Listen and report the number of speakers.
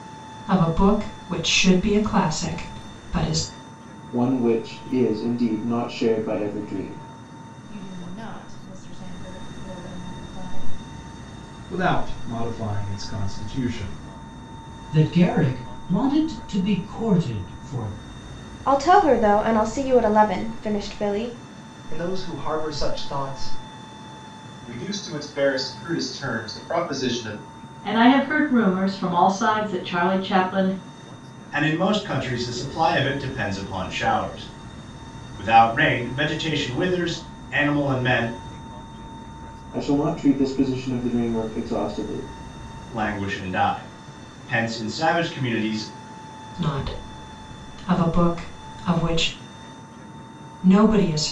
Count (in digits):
10